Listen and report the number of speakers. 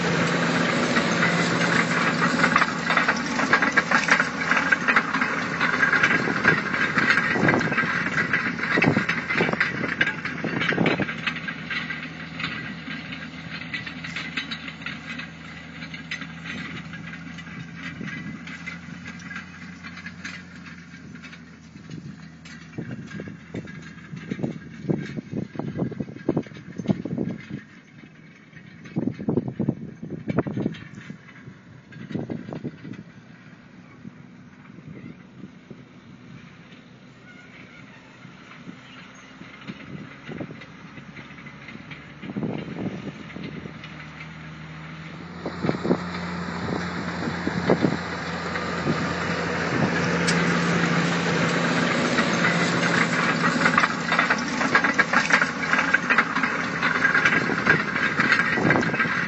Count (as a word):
zero